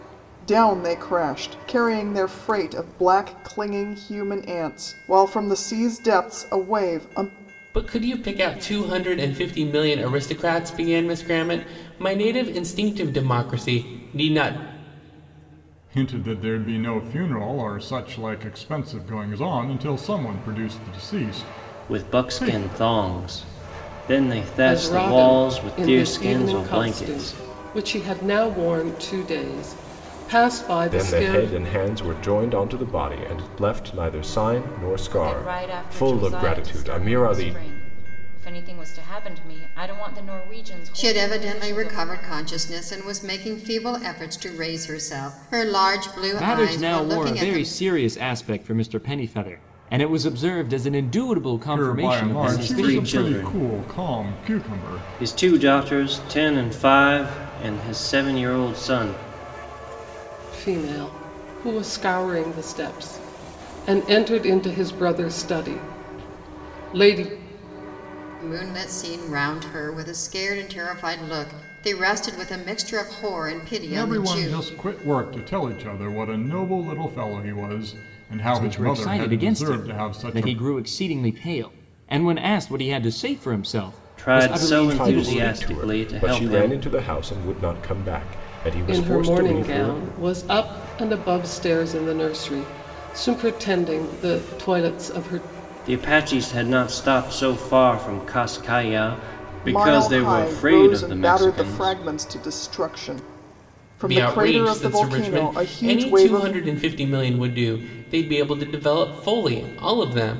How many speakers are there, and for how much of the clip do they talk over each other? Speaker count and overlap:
nine, about 22%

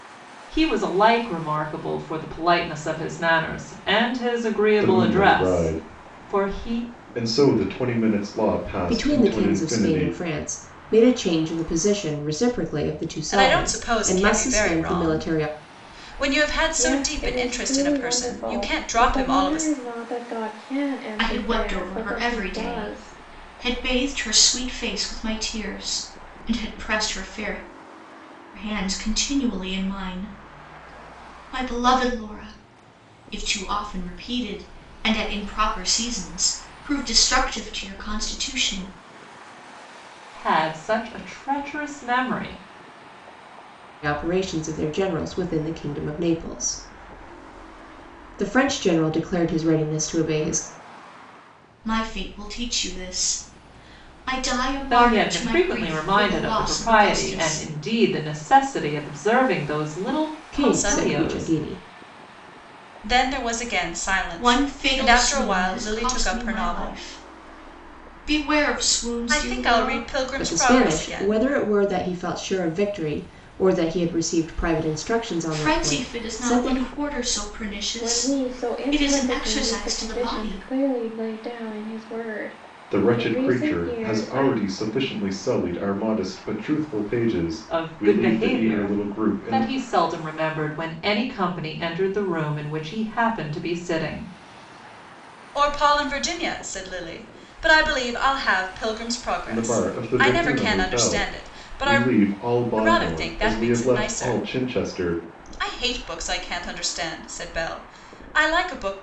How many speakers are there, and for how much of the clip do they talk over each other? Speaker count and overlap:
six, about 30%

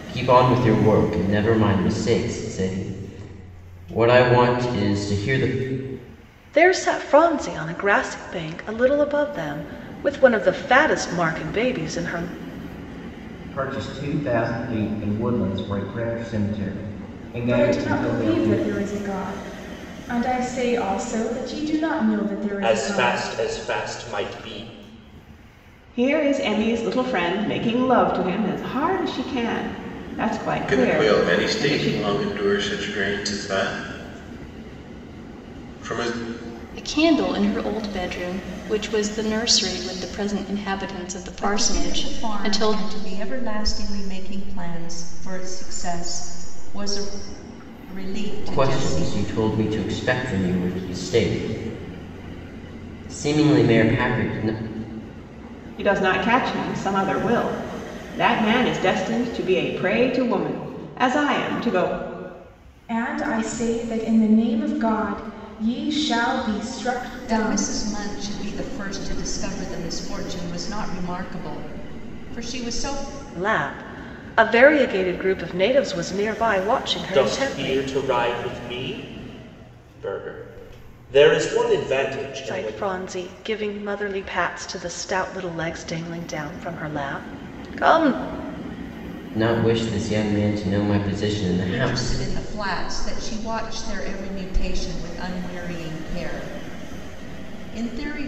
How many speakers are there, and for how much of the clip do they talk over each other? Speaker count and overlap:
nine, about 8%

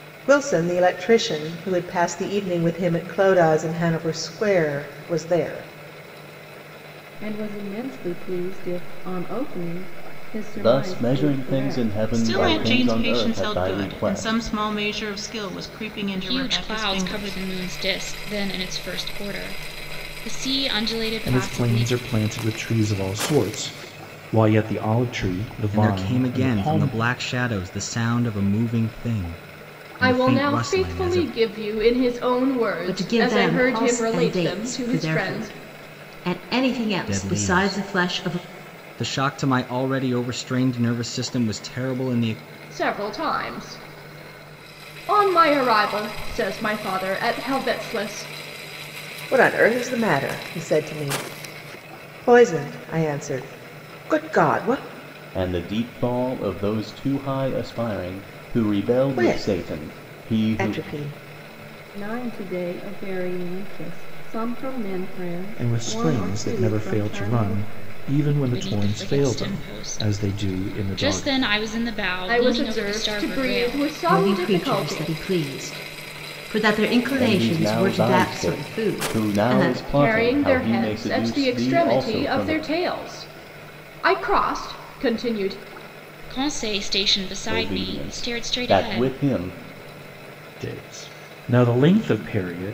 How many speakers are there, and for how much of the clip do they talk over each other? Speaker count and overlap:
nine, about 31%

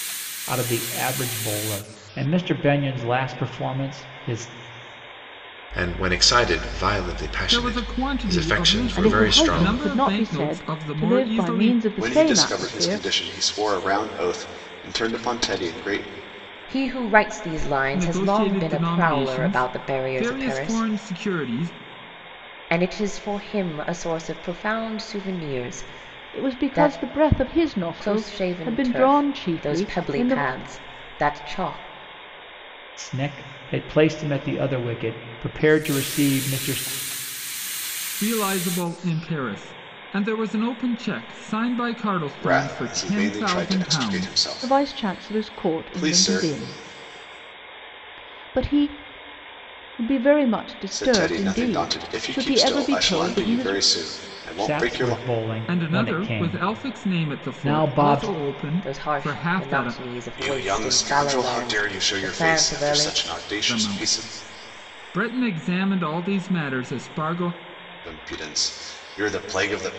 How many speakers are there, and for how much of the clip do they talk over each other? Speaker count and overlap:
six, about 38%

